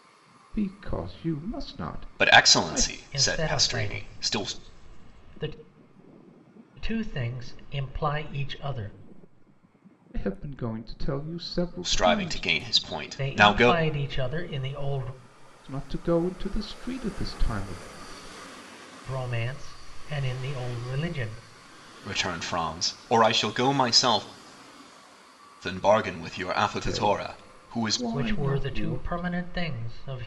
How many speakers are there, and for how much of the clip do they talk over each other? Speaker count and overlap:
three, about 19%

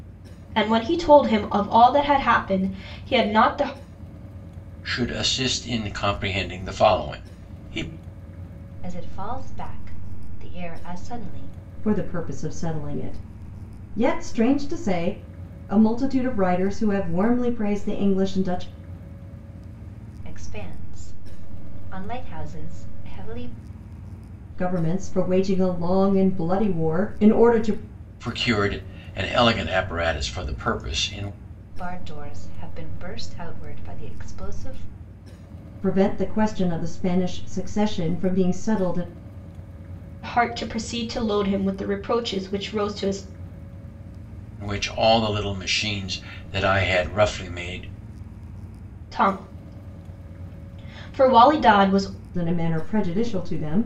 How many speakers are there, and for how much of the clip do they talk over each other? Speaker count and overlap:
four, no overlap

